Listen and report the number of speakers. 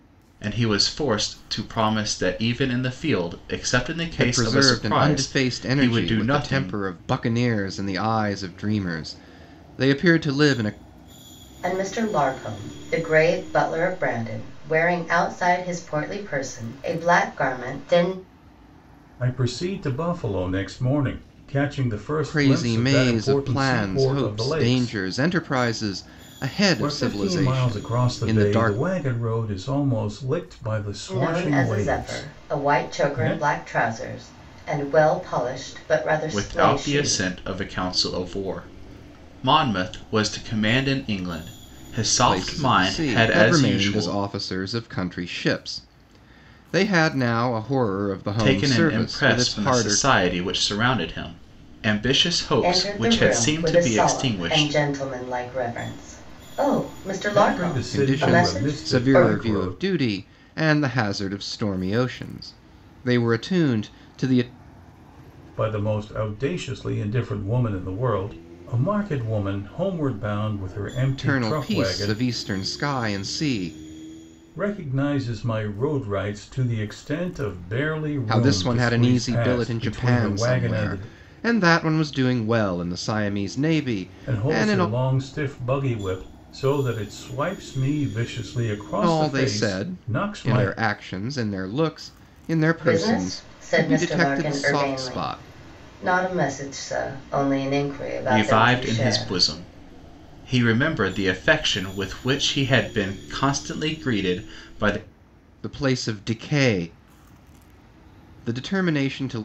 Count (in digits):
4